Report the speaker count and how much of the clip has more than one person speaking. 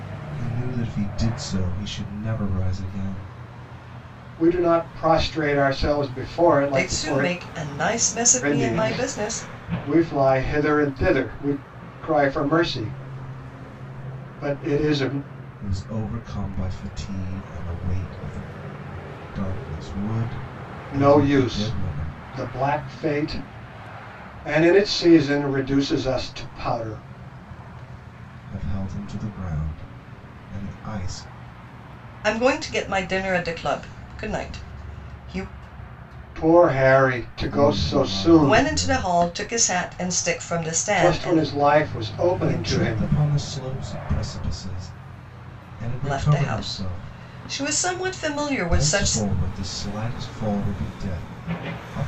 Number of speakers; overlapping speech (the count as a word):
three, about 15%